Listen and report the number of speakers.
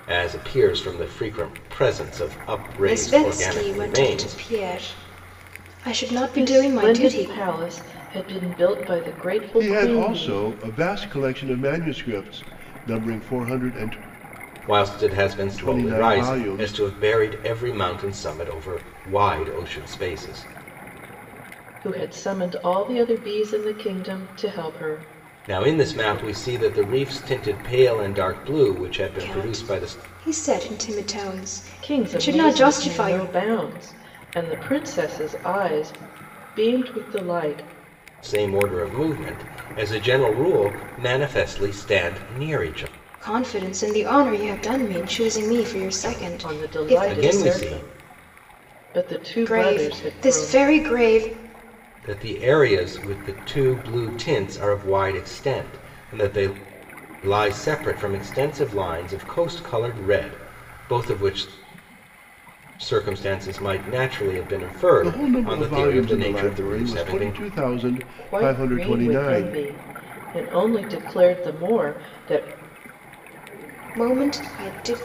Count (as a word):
four